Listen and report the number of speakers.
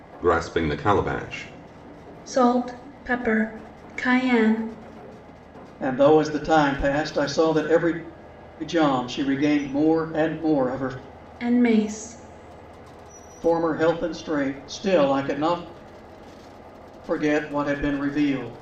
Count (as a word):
three